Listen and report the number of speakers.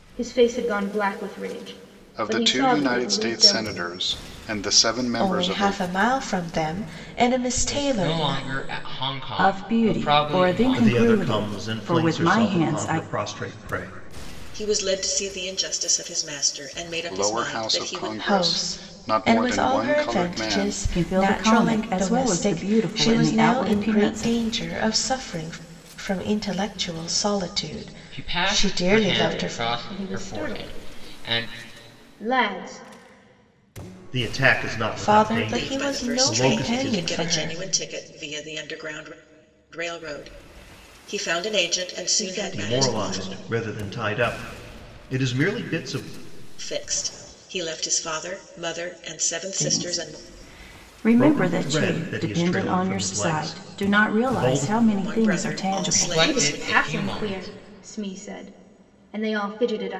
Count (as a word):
seven